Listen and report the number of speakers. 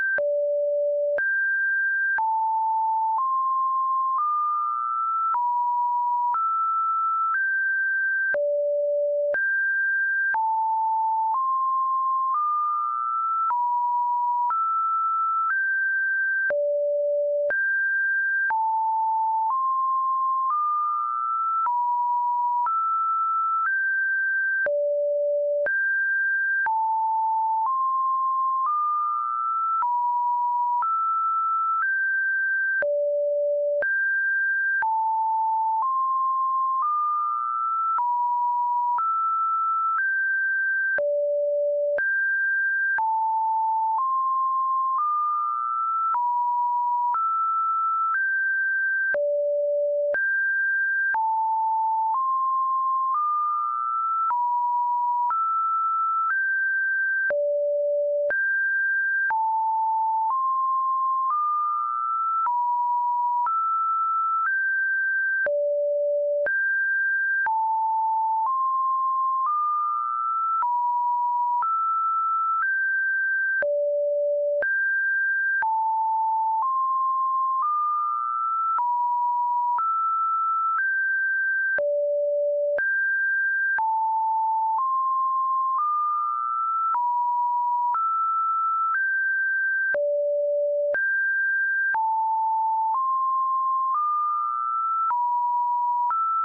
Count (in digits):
0